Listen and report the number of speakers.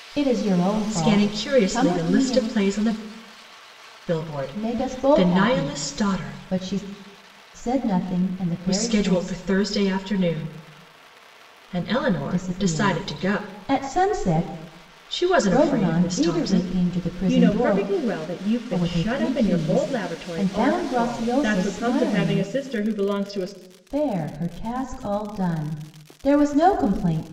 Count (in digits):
2